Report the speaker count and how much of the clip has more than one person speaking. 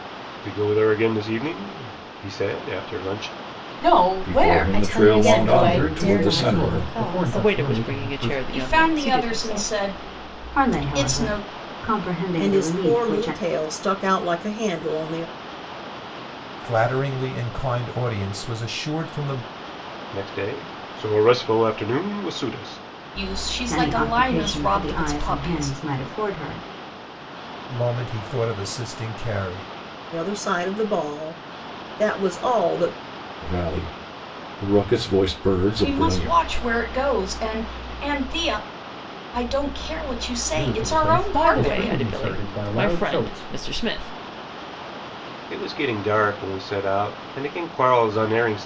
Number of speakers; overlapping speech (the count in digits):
10, about 27%